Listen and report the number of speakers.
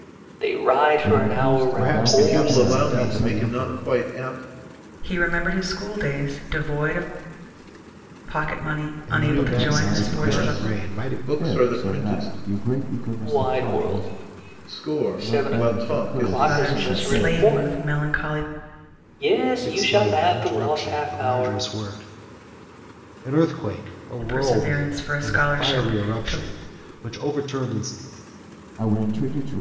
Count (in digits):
5